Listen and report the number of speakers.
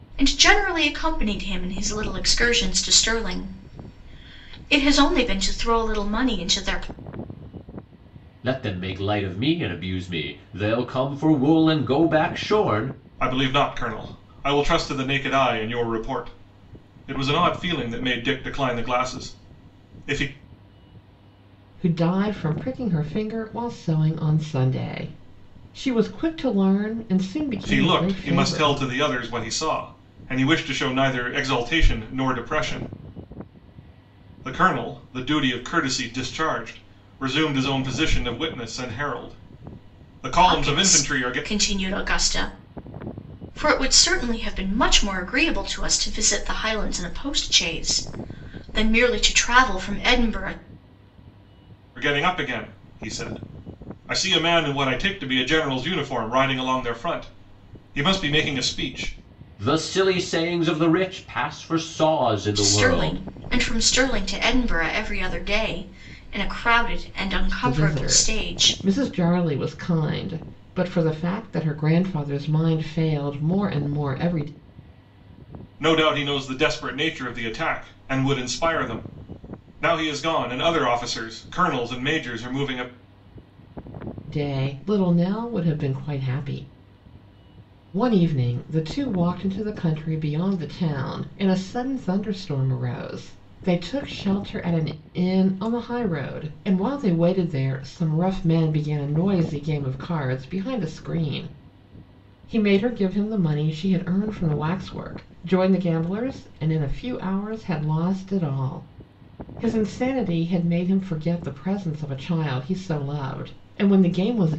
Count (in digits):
4